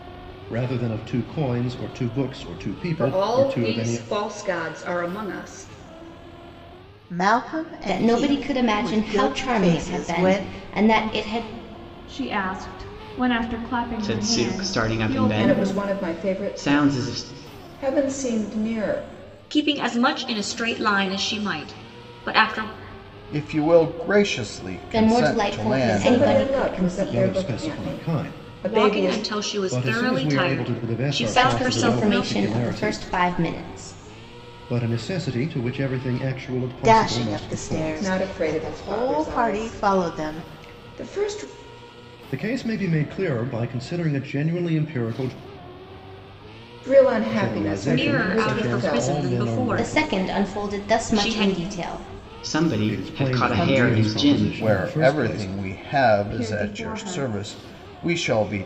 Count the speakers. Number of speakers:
nine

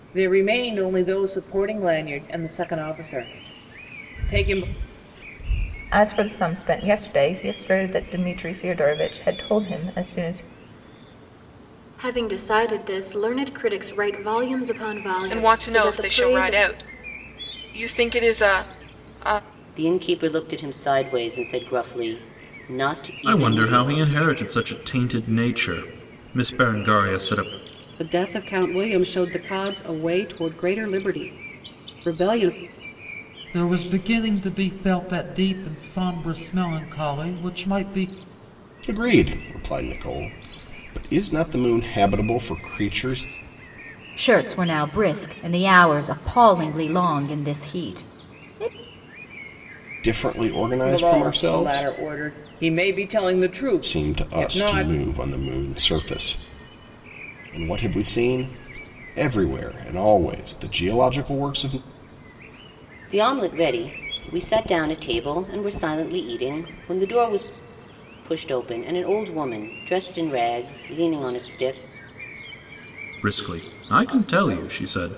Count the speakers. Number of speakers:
ten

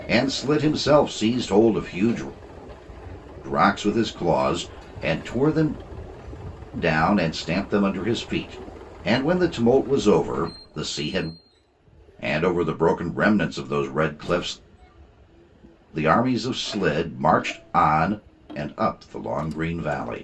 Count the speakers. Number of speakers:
one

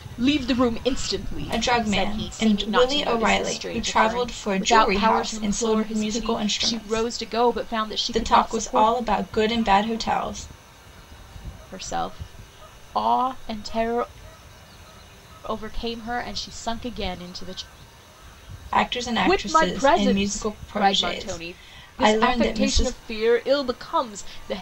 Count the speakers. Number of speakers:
two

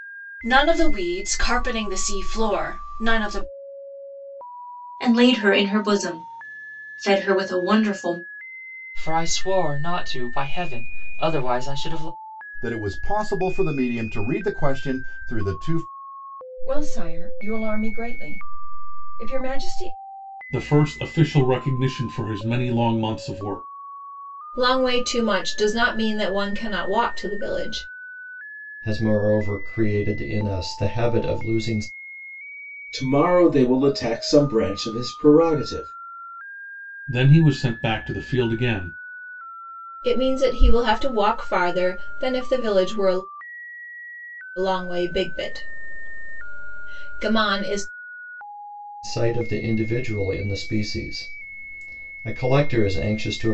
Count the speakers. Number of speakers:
nine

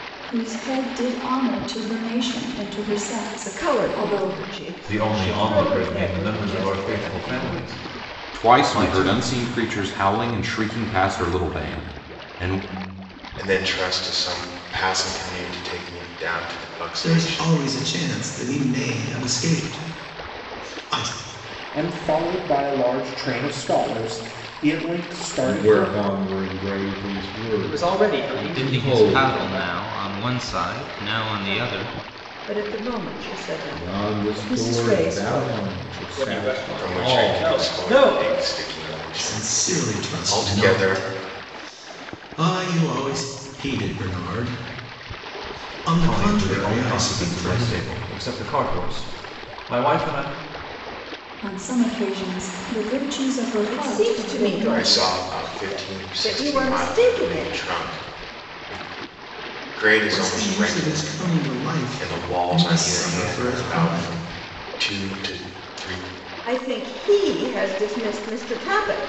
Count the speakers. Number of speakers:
ten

